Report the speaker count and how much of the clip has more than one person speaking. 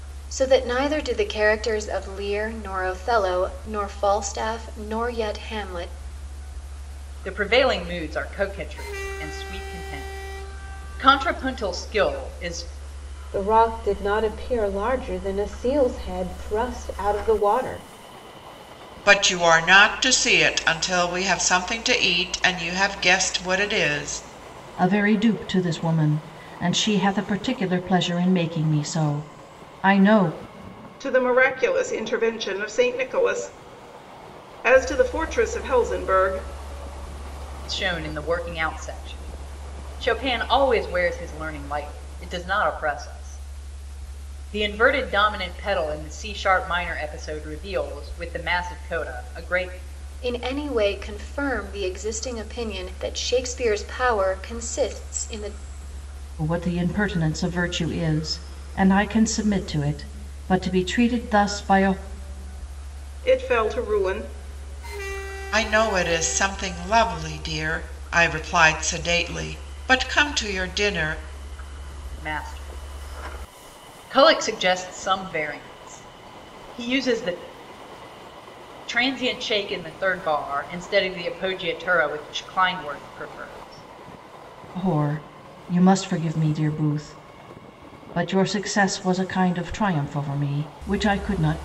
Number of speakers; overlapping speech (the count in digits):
6, no overlap